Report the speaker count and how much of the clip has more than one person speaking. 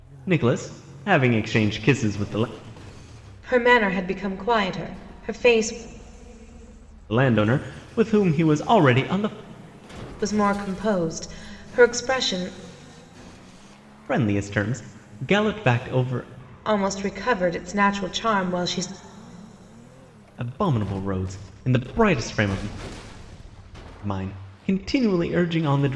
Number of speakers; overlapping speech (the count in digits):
2, no overlap